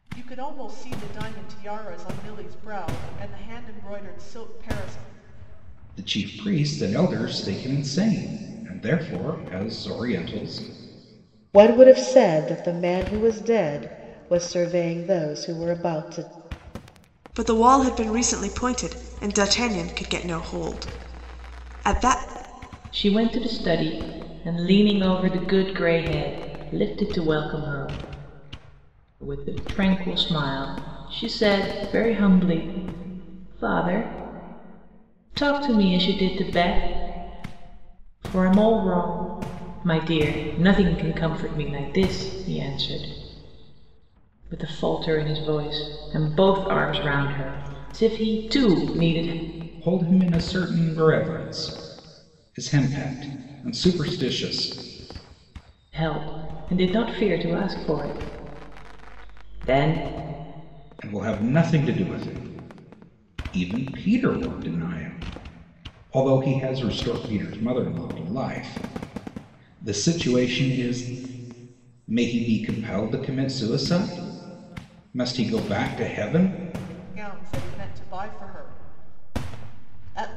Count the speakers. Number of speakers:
5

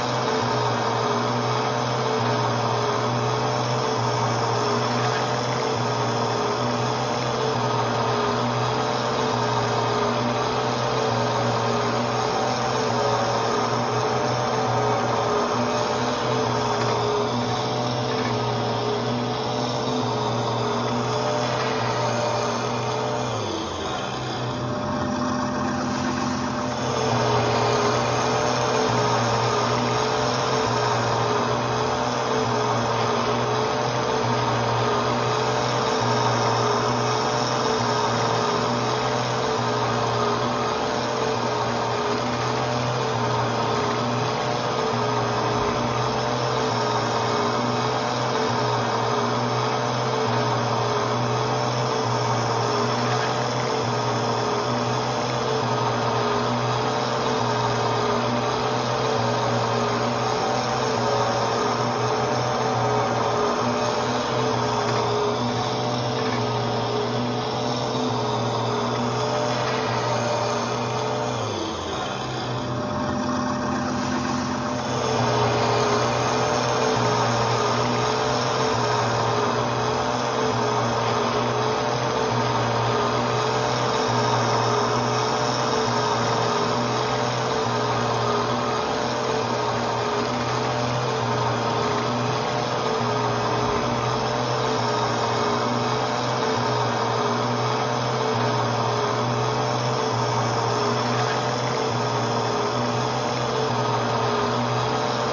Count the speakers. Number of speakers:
0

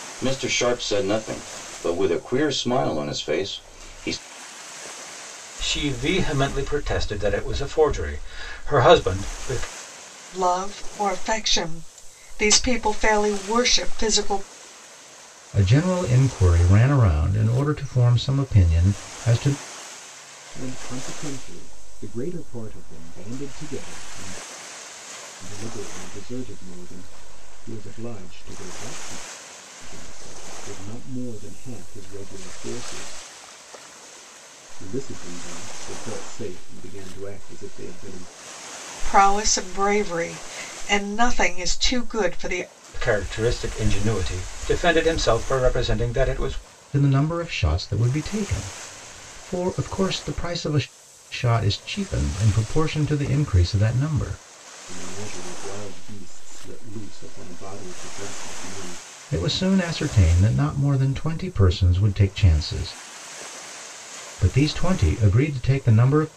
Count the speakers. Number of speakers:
5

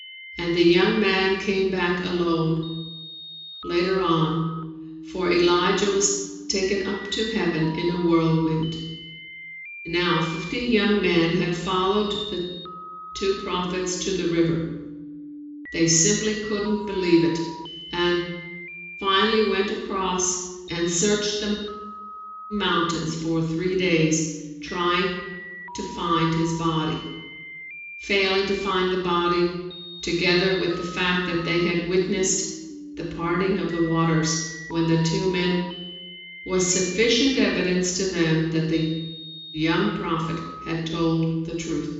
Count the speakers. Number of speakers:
1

